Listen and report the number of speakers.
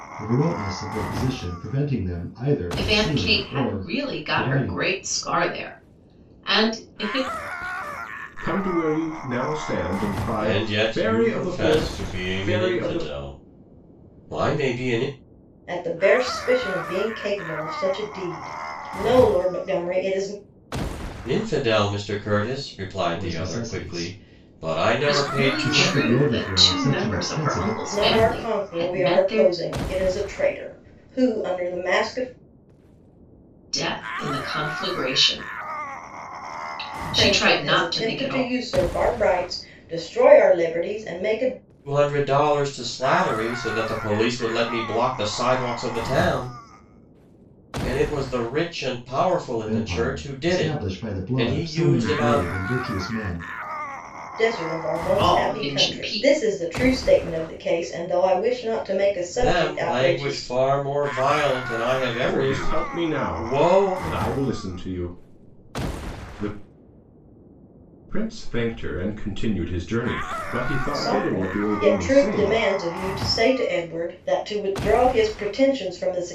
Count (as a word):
five